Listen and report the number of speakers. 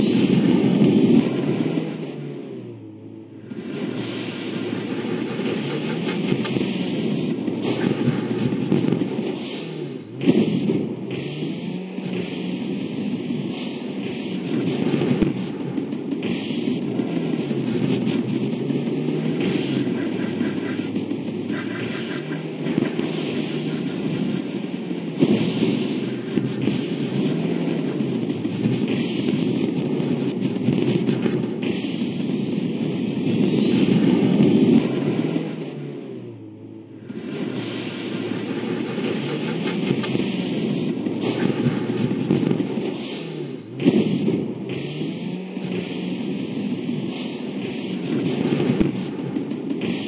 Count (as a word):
zero